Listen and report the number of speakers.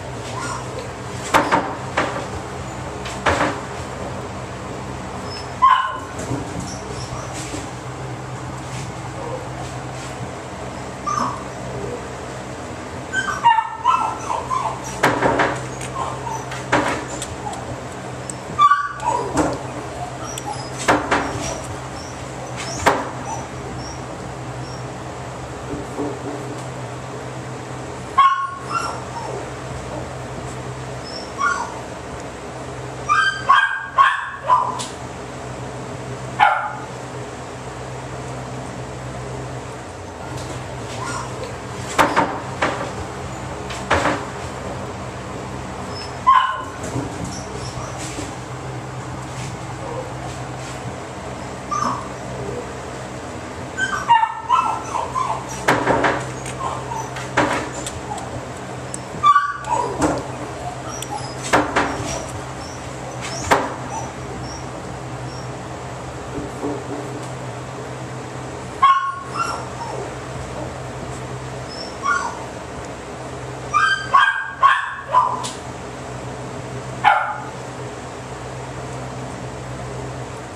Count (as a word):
zero